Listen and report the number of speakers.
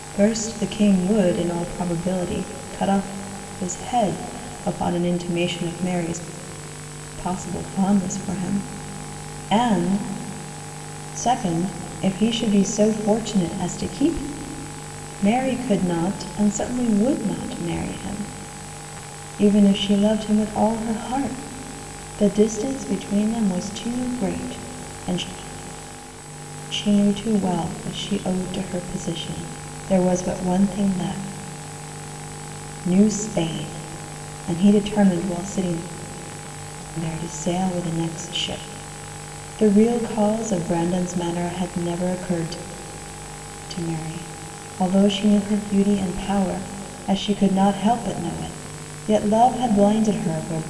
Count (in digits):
1